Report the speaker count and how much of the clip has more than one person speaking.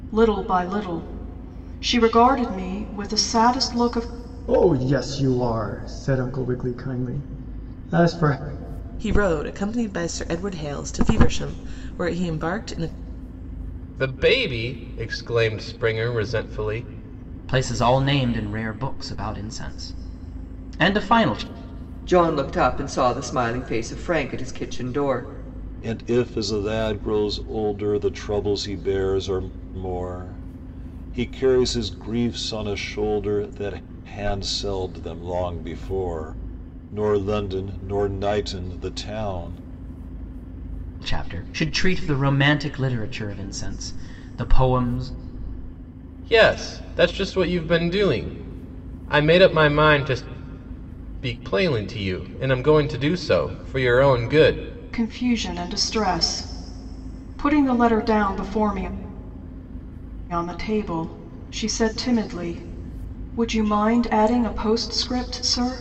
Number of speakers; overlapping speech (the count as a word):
seven, no overlap